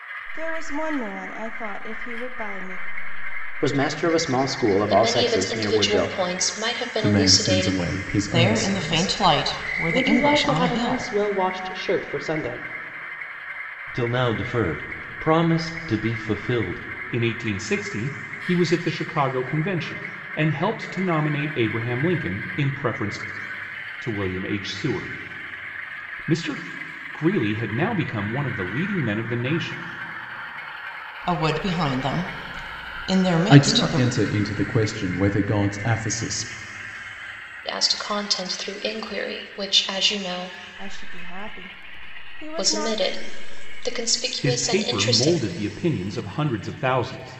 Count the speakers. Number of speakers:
eight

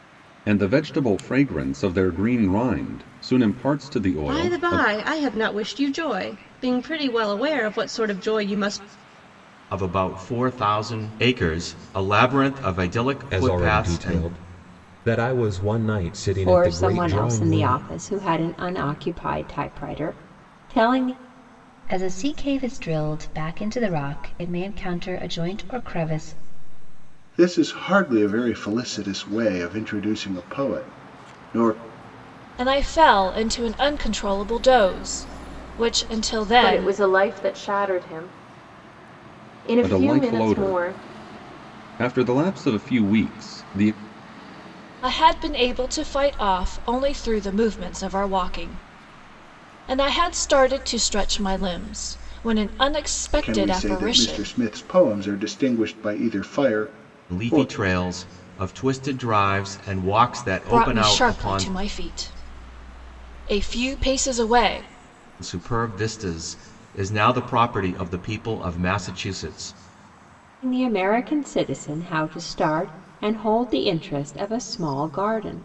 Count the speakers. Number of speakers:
nine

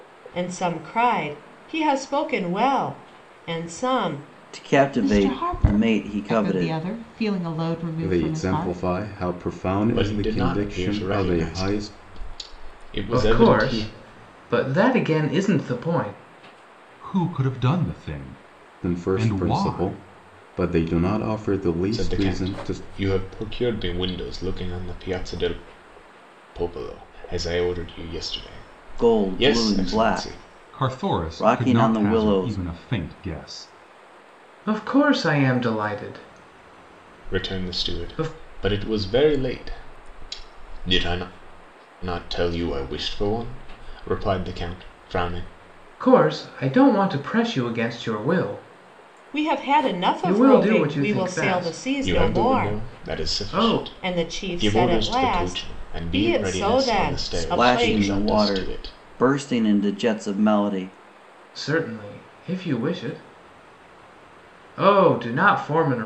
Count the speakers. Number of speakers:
seven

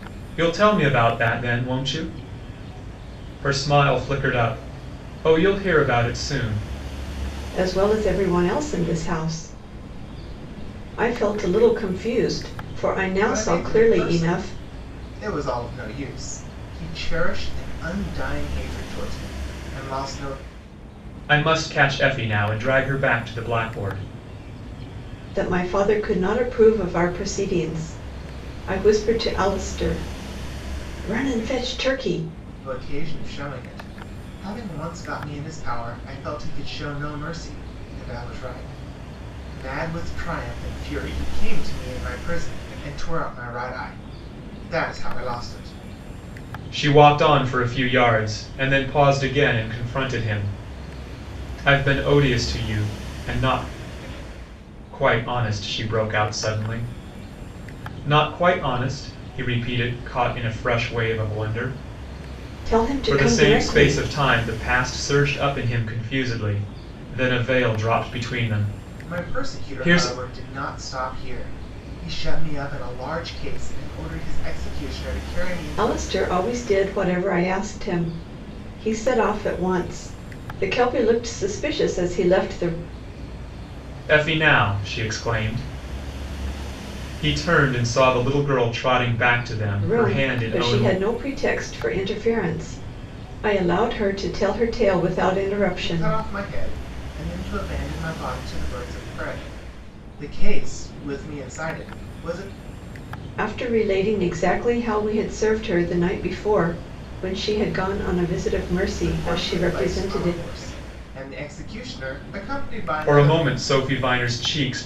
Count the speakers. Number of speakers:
three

